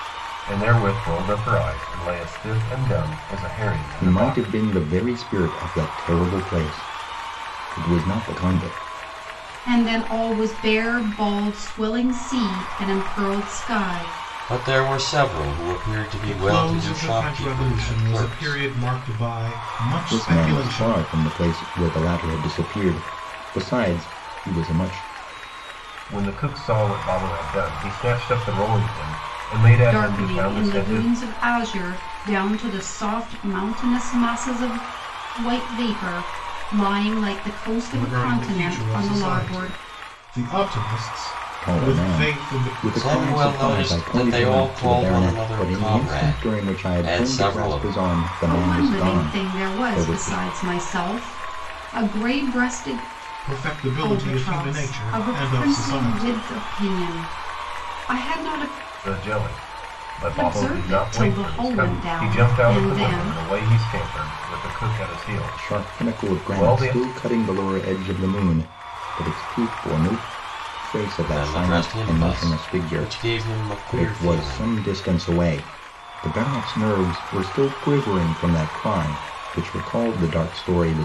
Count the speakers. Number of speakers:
5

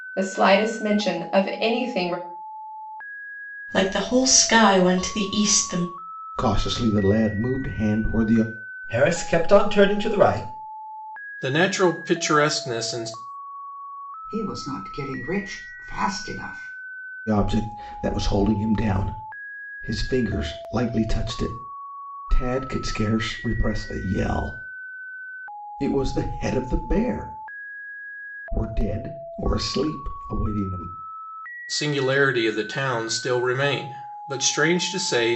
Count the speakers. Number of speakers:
6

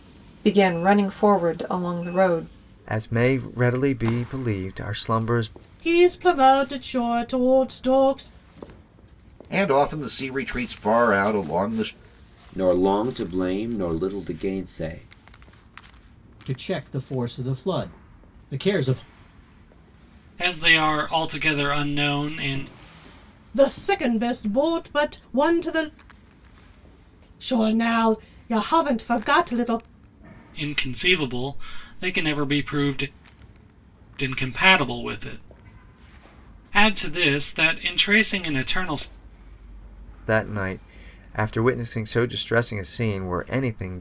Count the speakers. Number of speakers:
7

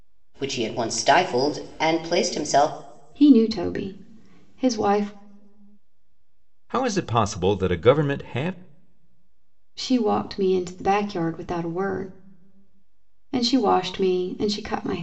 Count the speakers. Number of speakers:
3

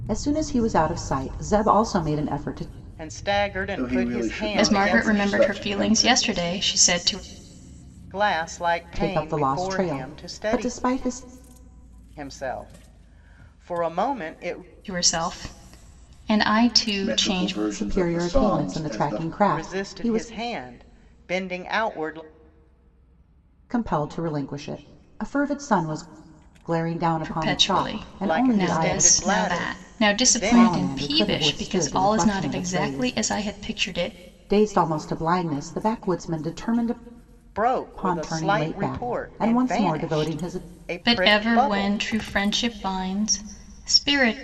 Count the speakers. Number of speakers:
4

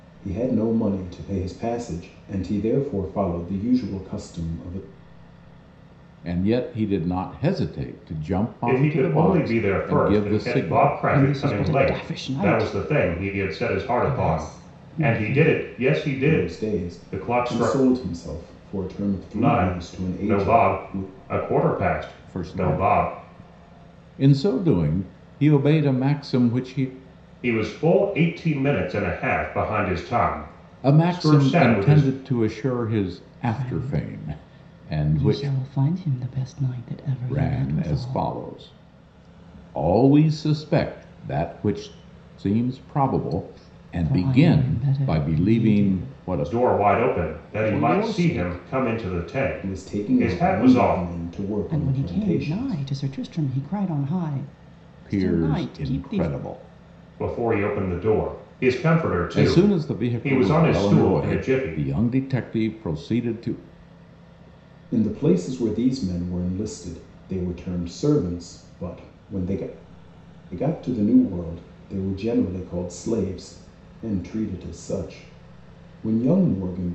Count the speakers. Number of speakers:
4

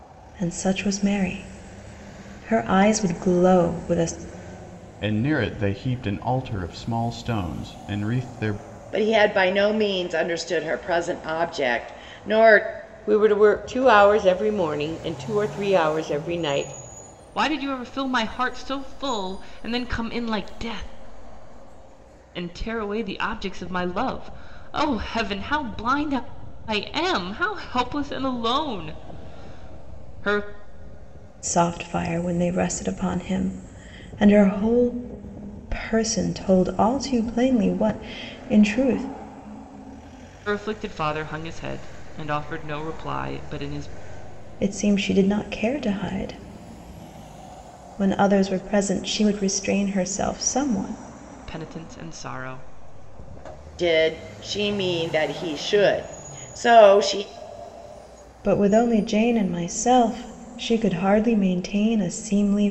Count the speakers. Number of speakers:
5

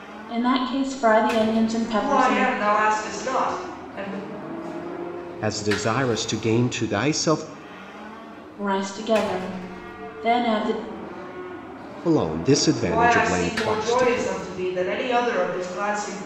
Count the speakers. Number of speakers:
3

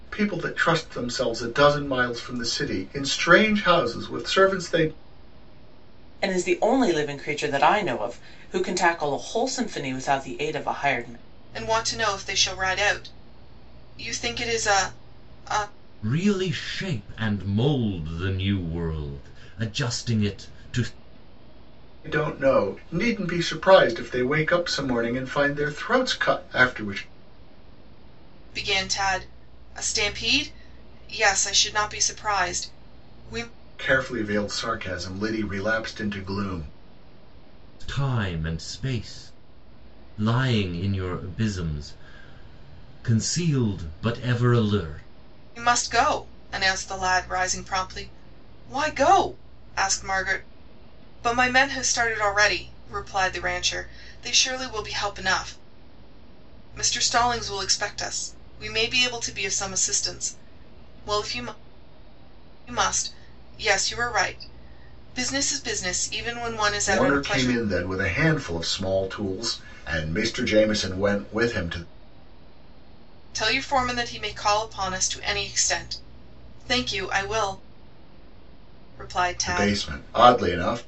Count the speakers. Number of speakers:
4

